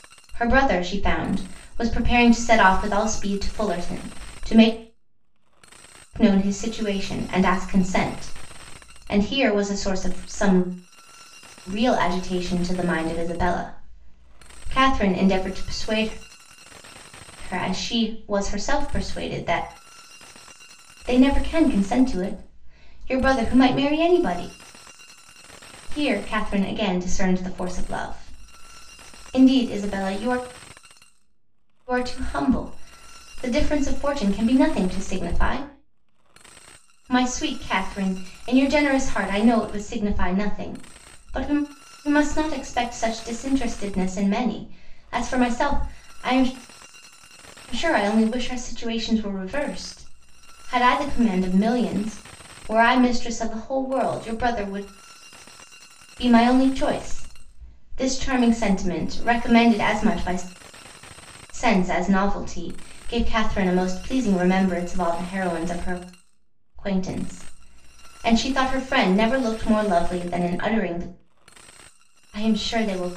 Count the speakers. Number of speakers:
1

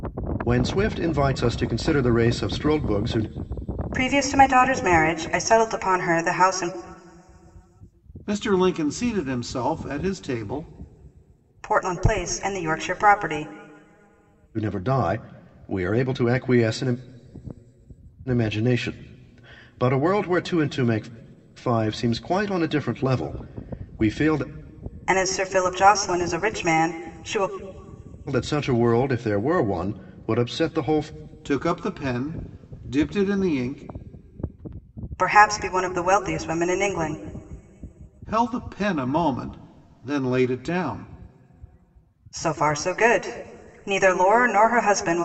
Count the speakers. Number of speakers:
3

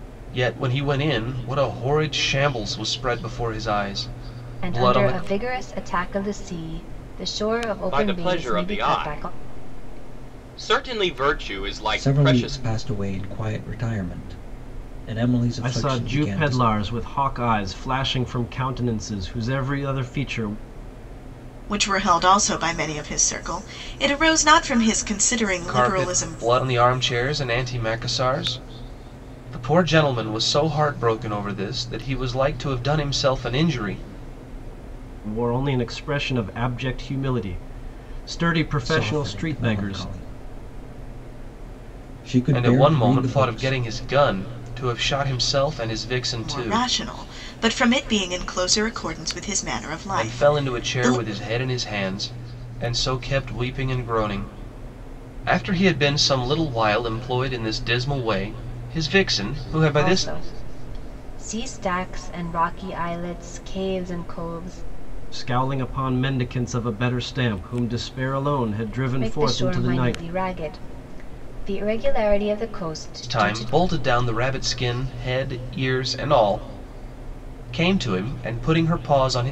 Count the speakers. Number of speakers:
6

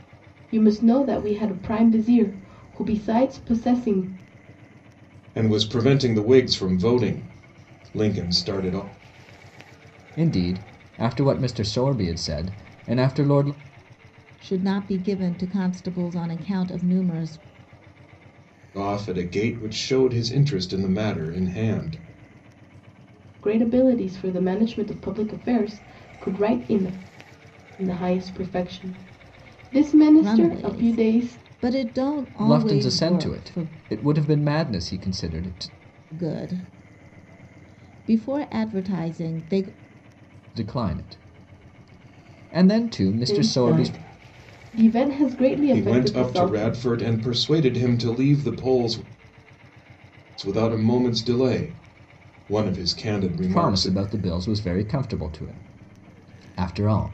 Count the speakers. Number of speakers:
4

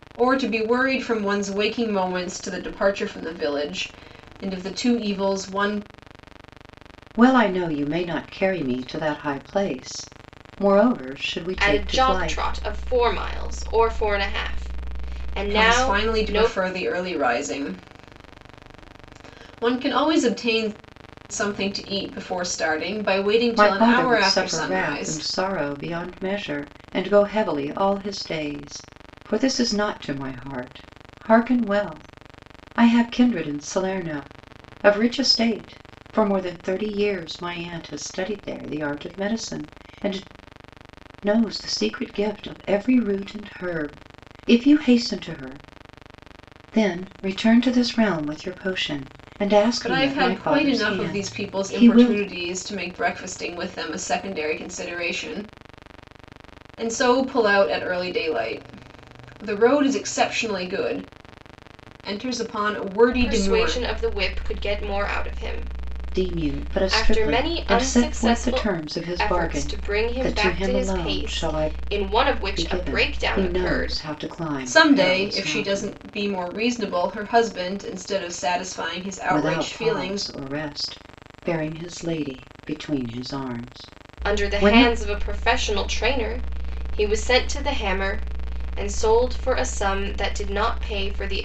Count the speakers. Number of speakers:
3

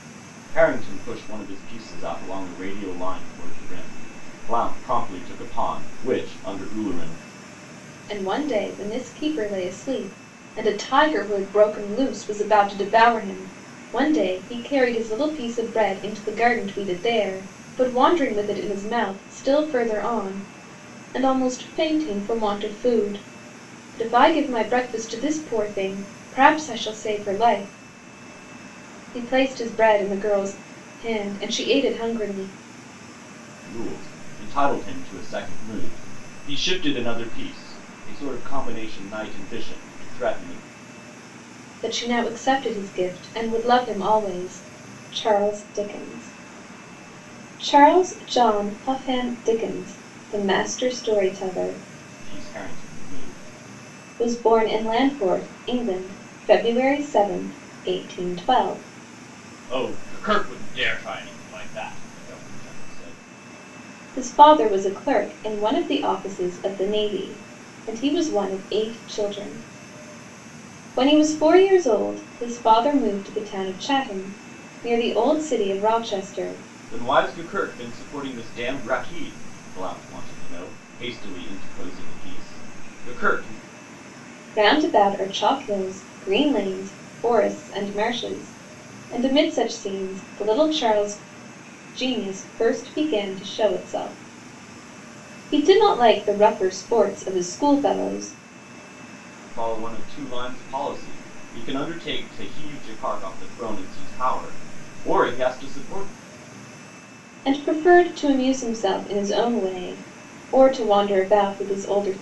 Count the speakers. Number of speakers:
2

